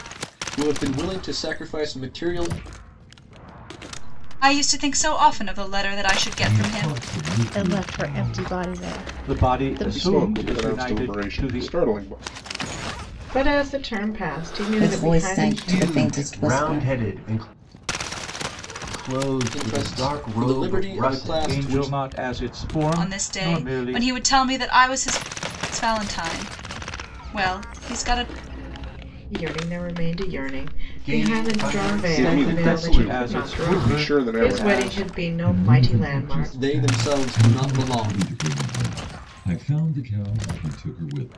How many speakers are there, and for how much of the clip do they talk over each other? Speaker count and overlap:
ten, about 47%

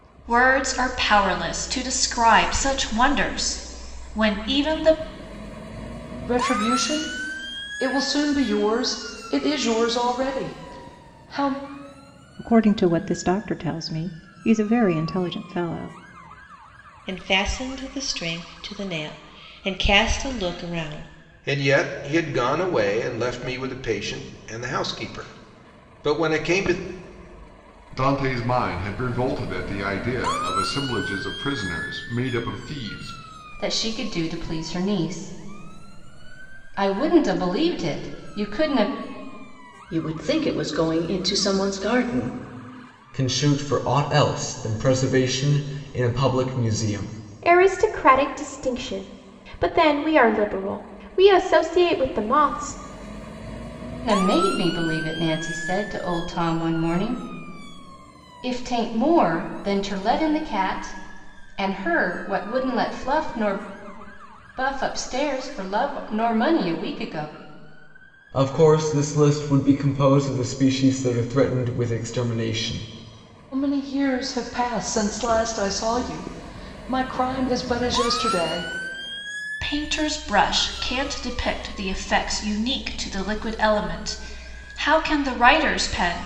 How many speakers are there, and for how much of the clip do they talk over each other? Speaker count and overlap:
ten, no overlap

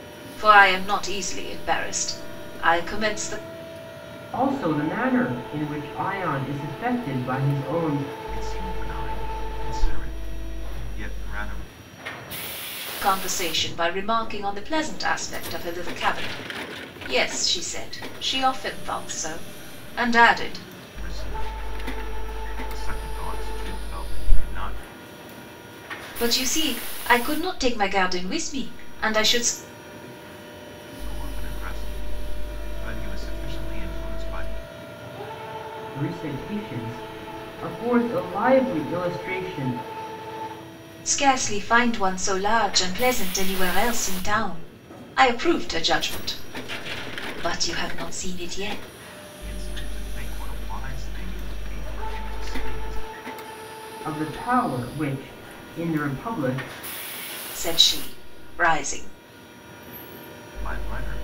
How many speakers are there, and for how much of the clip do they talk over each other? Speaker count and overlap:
three, no overlap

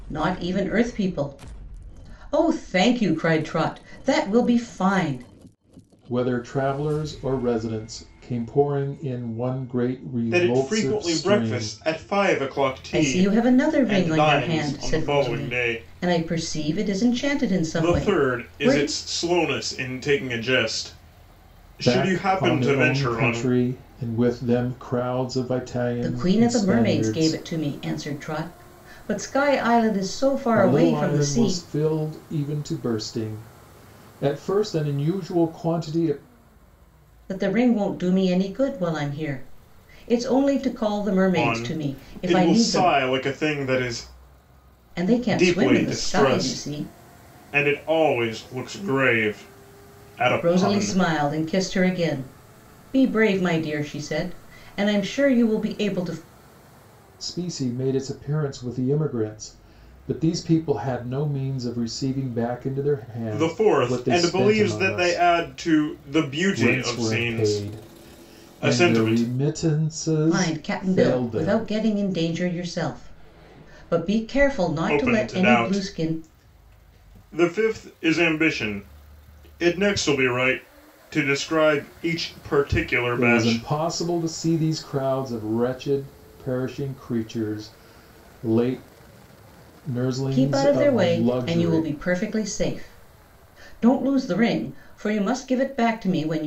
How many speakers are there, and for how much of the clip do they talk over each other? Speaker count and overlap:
three, about 26%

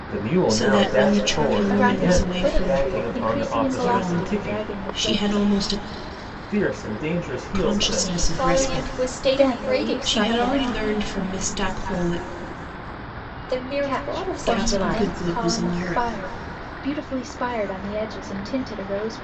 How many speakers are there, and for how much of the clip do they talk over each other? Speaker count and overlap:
four, about 55%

